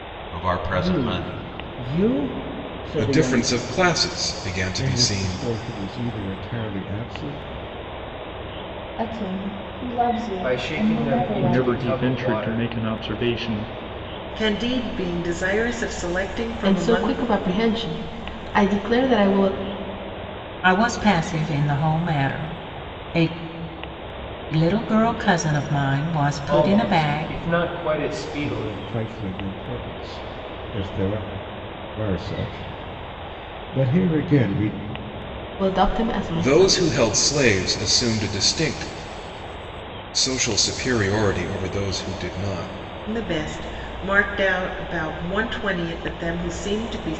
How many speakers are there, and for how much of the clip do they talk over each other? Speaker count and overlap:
ten, about 14%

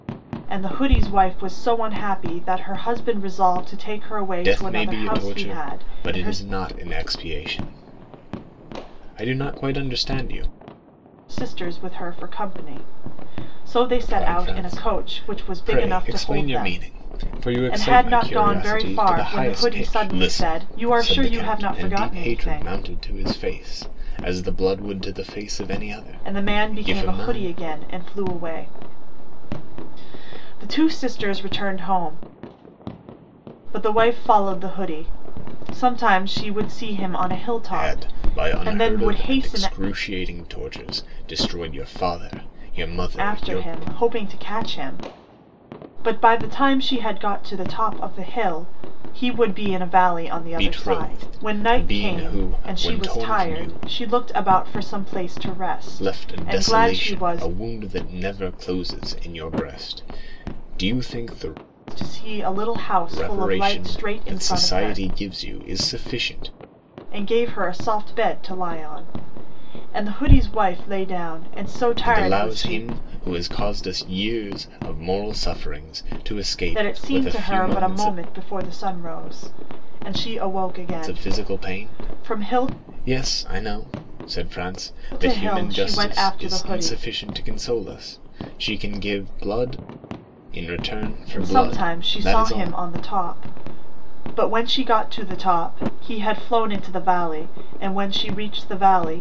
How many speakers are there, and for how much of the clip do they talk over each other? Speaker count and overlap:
two, about 28%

